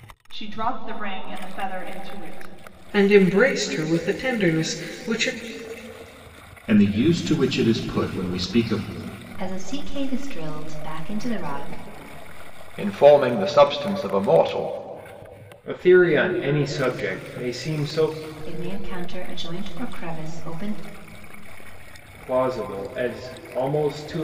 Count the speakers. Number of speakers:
6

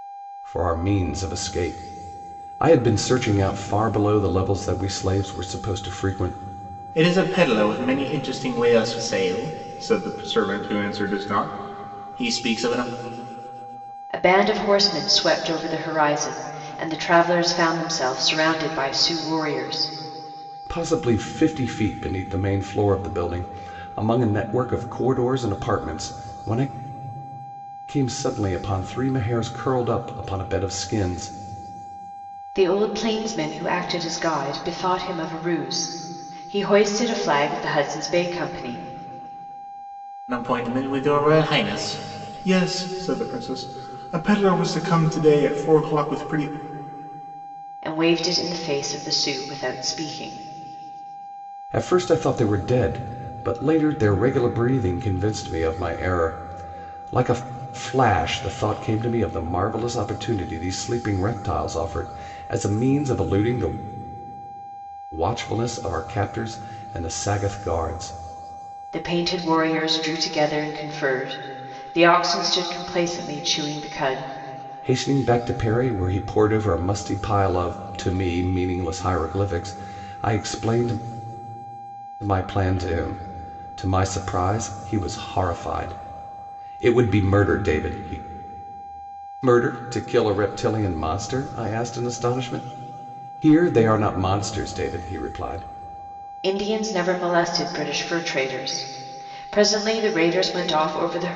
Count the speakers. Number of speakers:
3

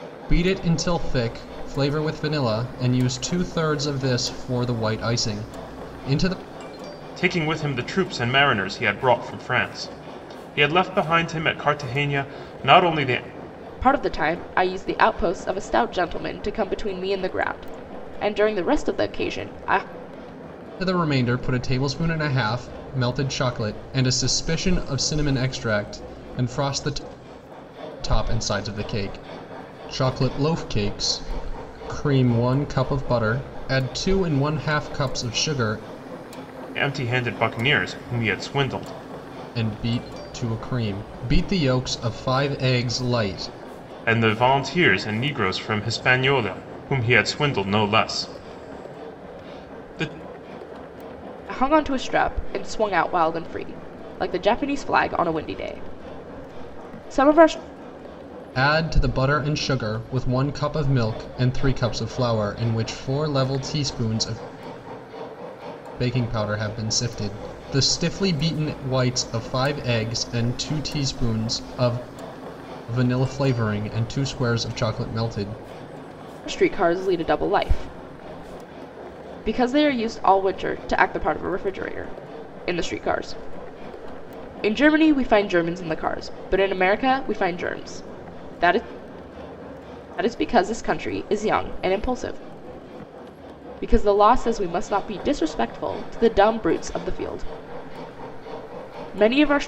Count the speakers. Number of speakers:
3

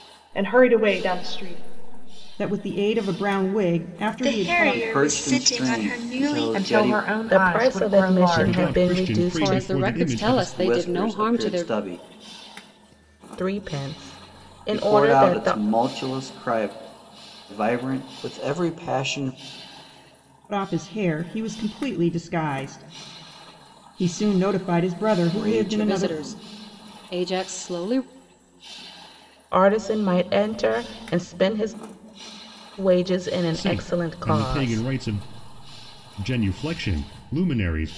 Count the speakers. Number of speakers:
8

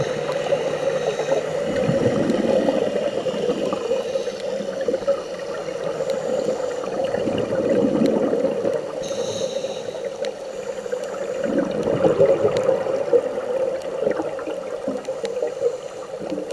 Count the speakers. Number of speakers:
0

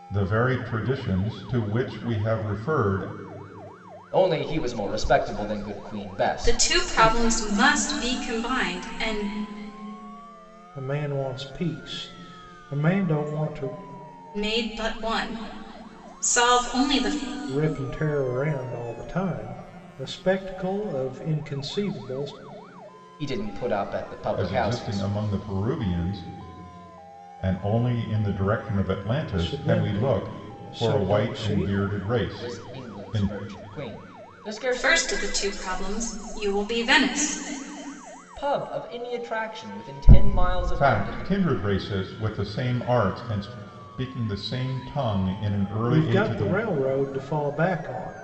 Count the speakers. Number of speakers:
4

